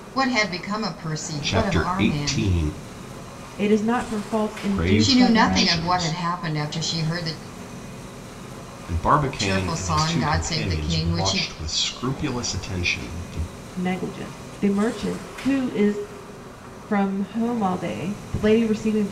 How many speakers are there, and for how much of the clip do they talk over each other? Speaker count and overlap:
three, about 25%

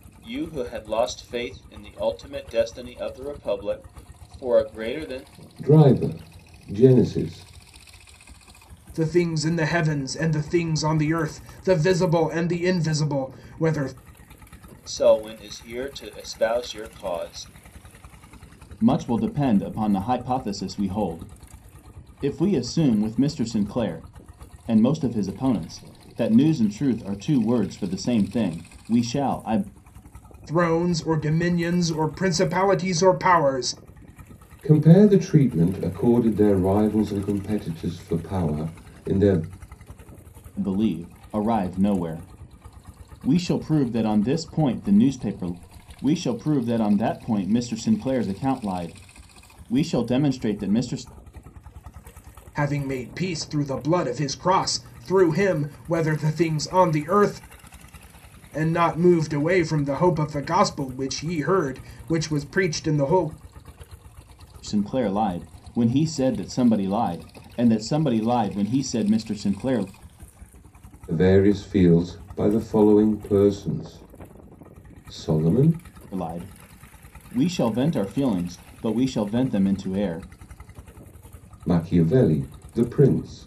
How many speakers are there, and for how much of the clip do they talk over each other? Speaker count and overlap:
three, no overlap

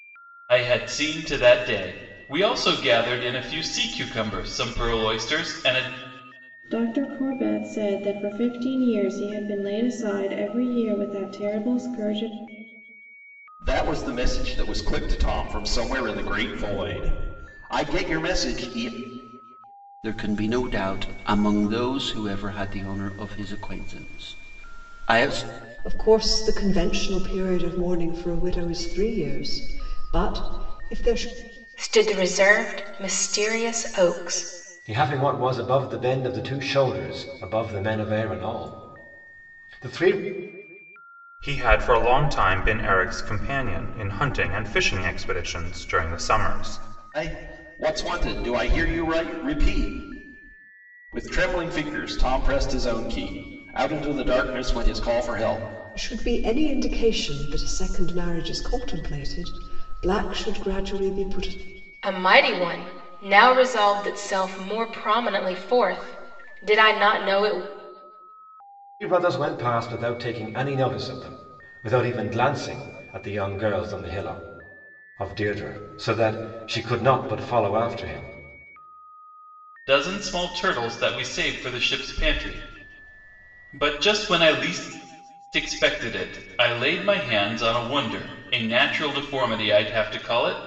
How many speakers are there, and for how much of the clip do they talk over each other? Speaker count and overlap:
eight, no overlap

